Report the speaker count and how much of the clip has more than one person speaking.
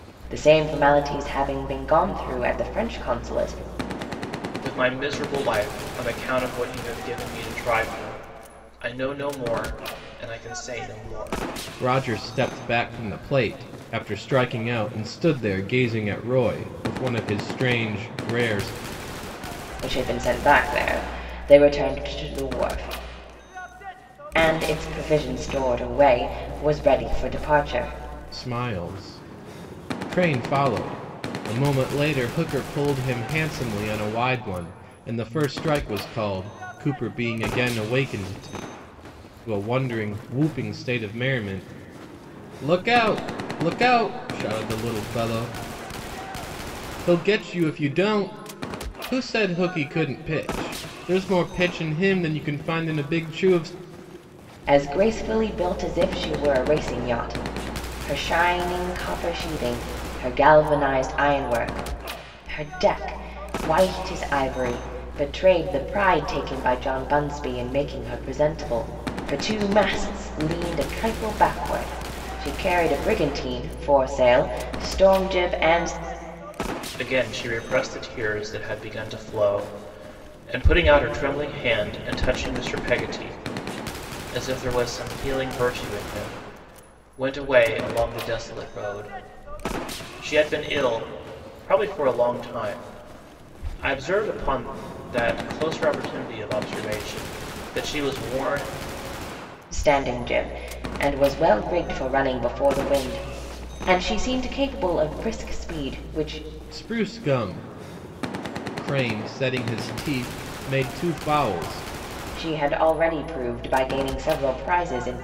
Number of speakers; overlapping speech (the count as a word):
three, no overlap